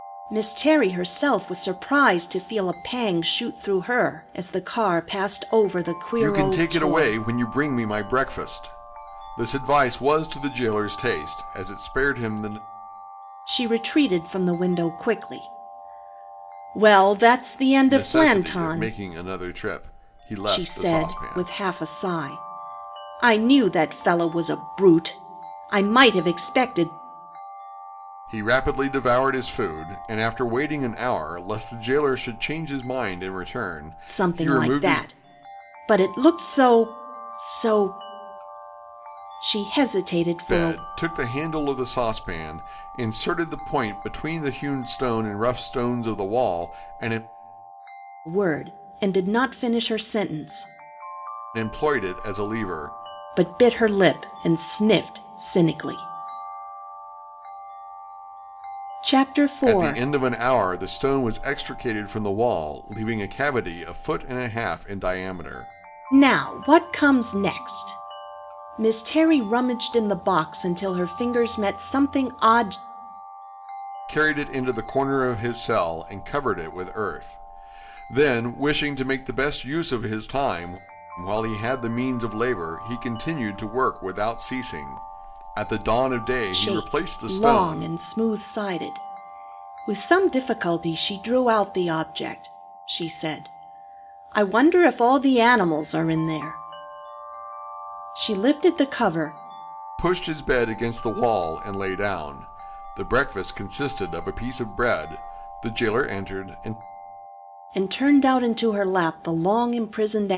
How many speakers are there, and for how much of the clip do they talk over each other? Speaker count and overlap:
2, about 6%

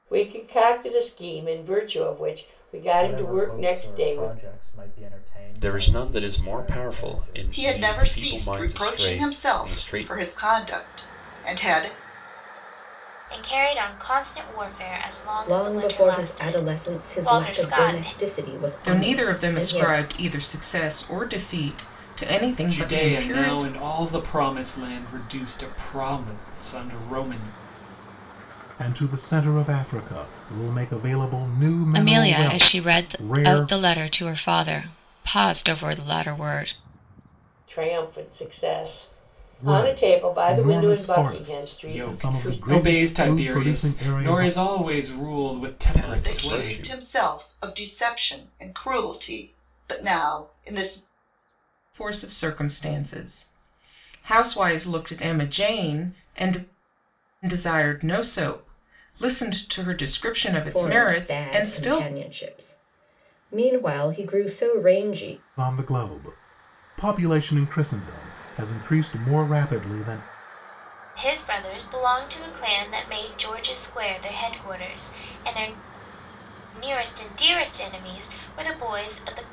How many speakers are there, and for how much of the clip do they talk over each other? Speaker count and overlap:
10, about 26%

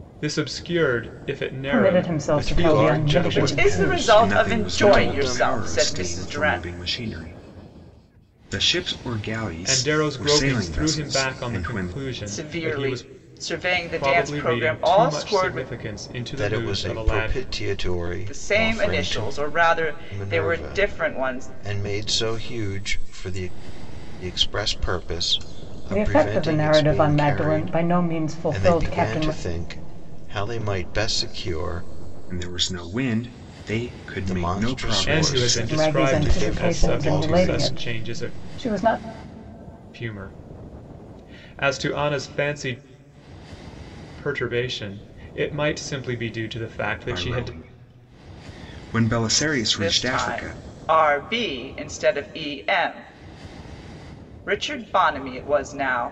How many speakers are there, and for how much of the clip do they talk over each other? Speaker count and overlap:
5, about 40%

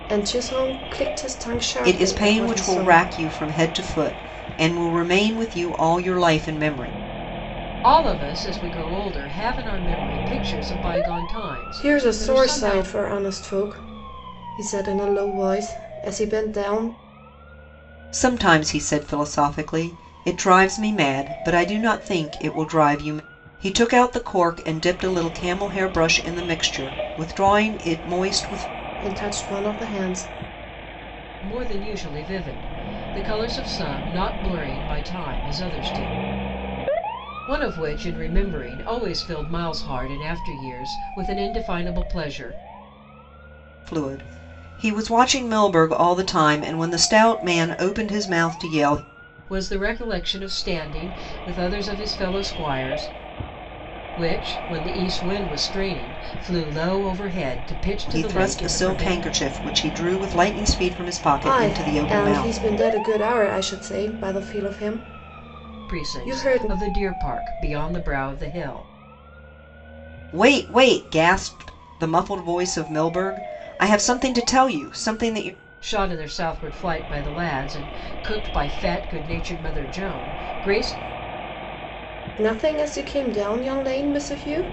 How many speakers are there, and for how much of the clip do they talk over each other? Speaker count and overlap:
3, about 7%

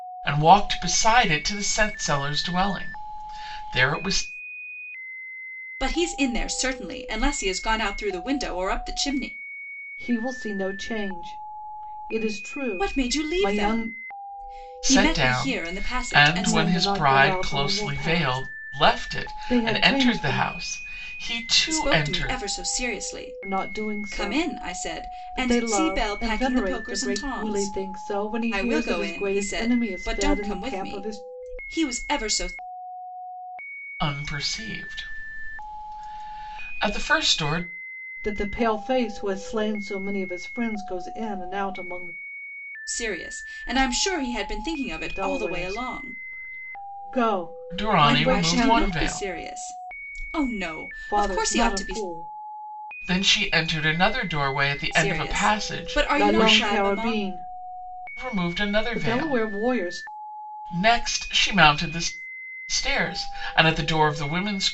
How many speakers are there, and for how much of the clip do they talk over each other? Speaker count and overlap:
3, about 34%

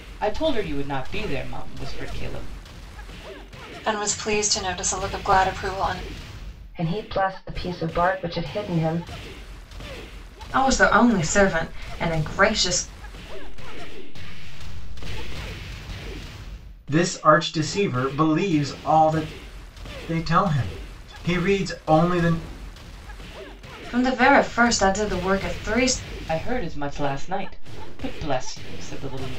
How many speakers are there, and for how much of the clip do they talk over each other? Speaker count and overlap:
6, no overlap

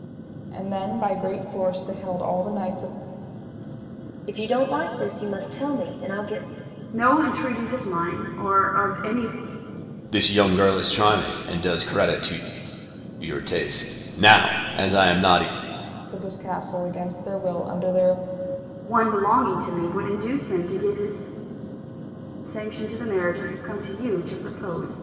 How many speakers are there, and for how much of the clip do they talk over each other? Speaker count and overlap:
4, no overlap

